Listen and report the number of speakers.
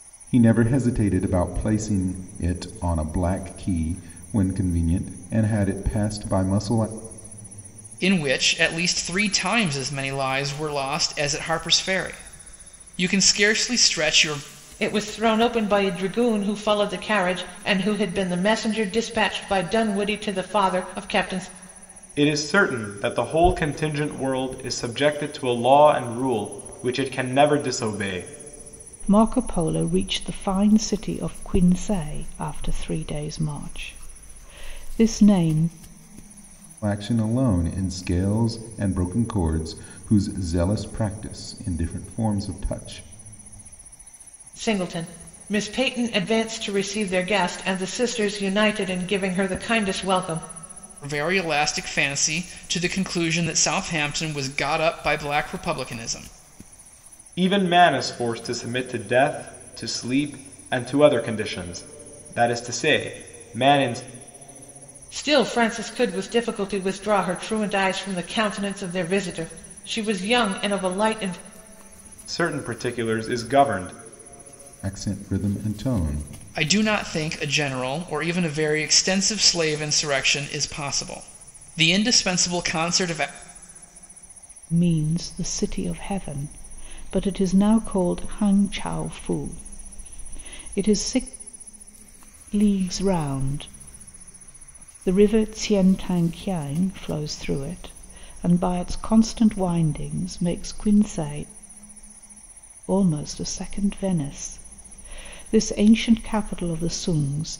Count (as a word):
five